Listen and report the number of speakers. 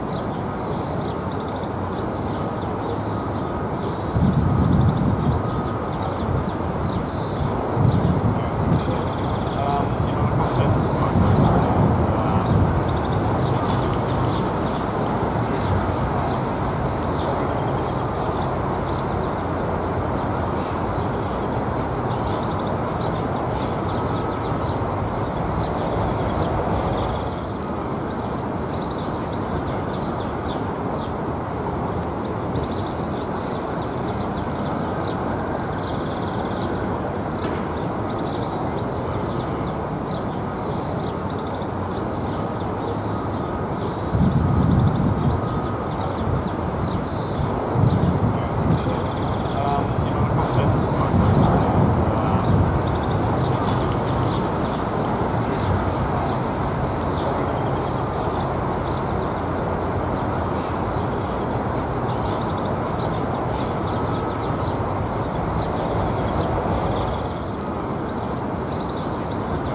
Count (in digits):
0